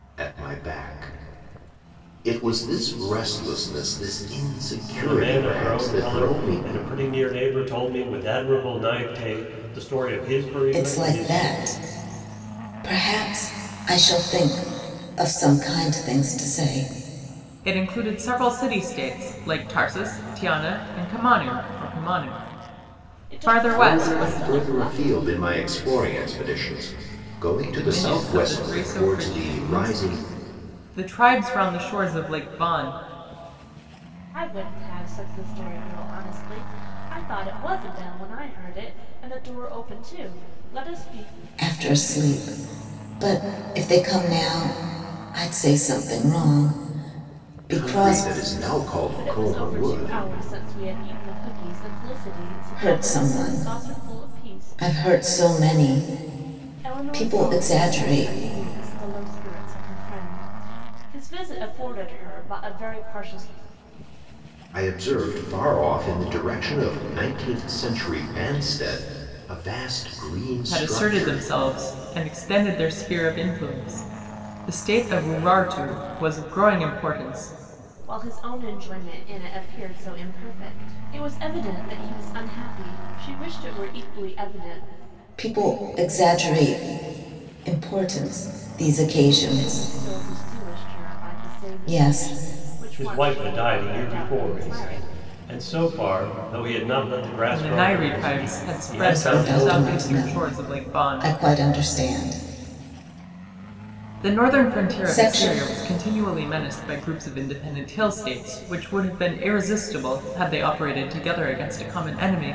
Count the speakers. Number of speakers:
5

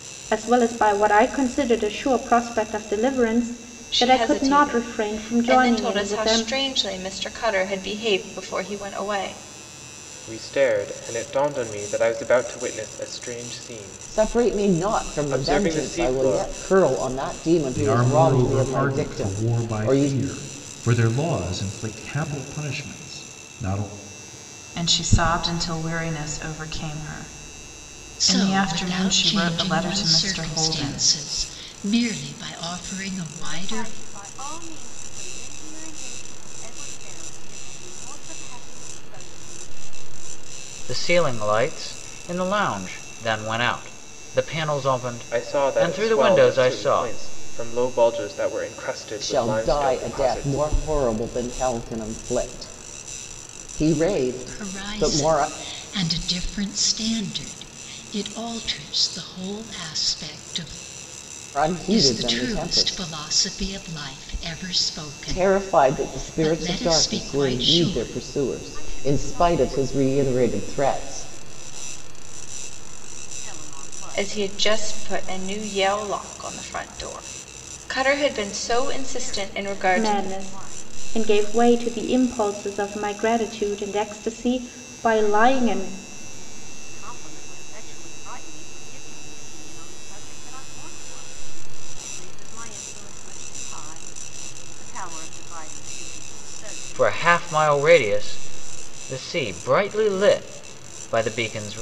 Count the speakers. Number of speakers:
9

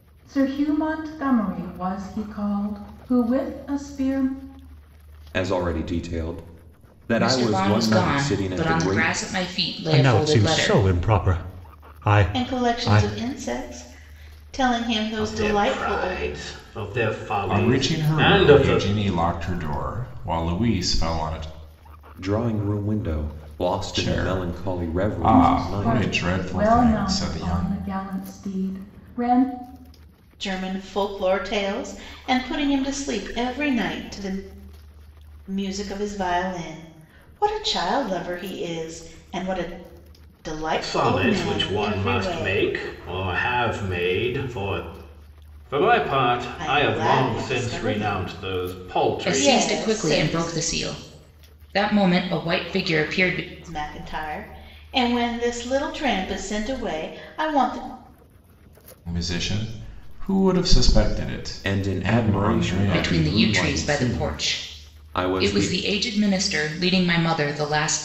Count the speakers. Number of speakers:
7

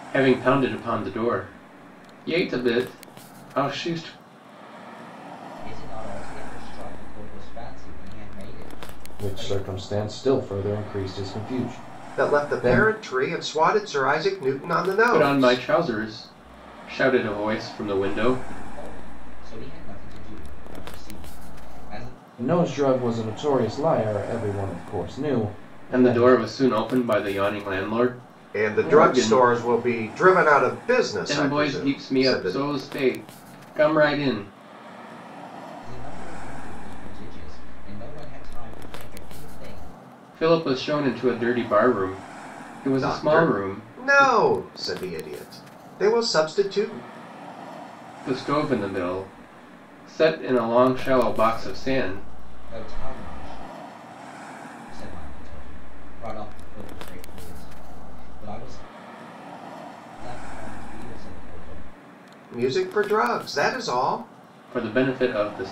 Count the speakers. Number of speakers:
4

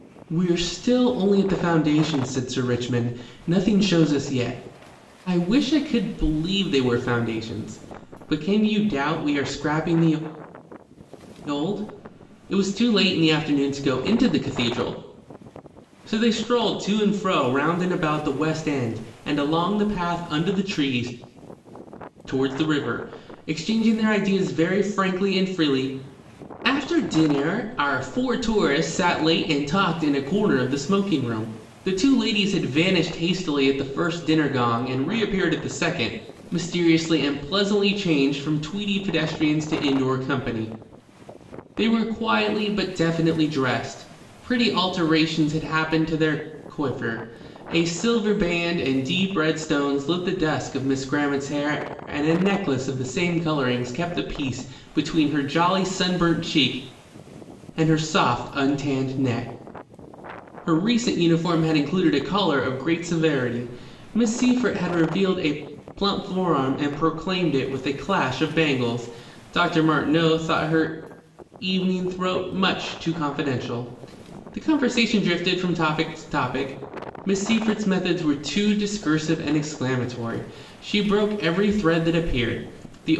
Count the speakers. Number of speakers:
1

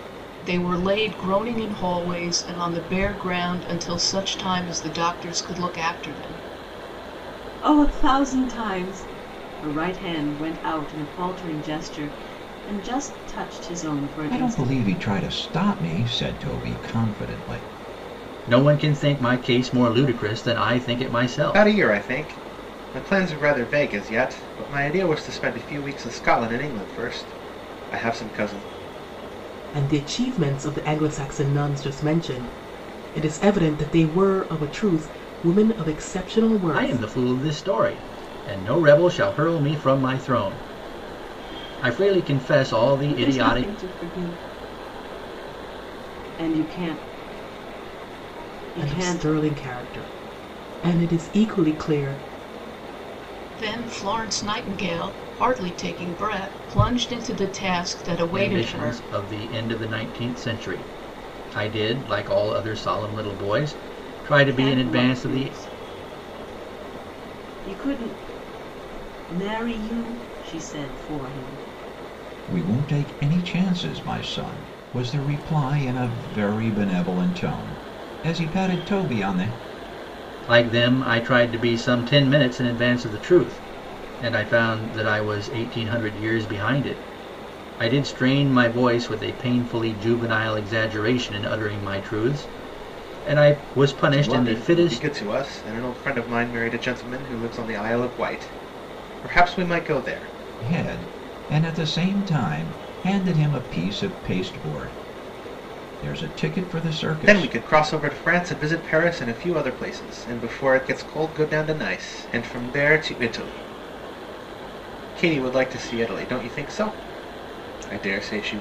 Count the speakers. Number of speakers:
6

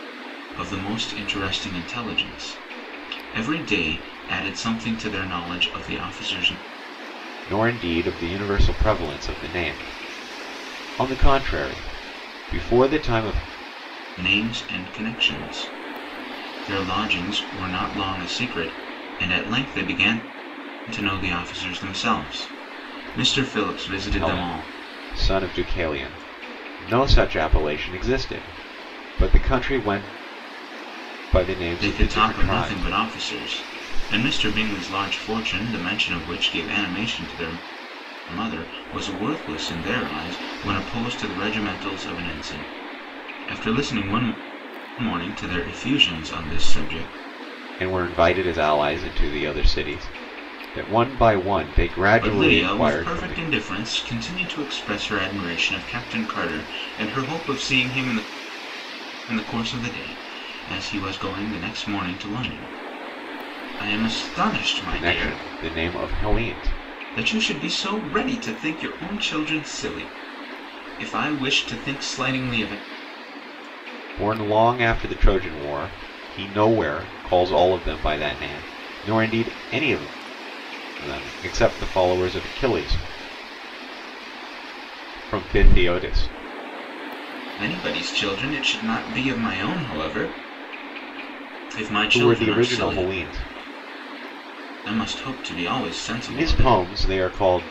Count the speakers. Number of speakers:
2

